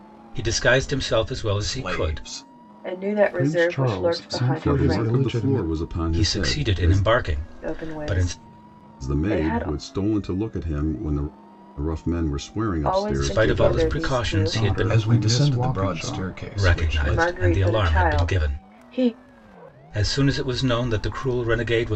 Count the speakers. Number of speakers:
5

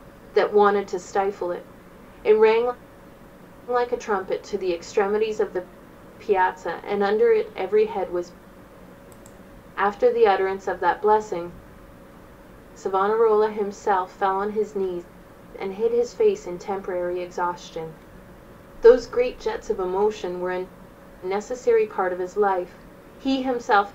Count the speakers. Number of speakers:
1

